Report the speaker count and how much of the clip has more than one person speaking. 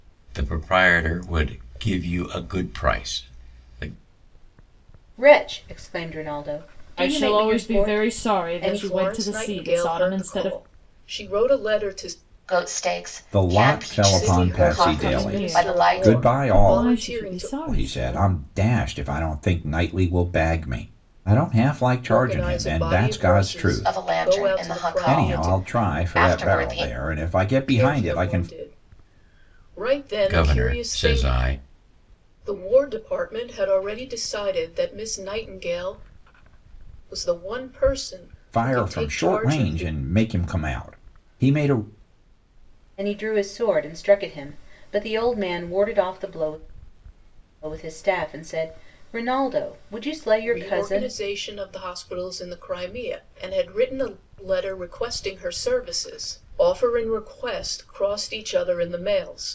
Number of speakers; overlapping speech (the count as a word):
six, about 29%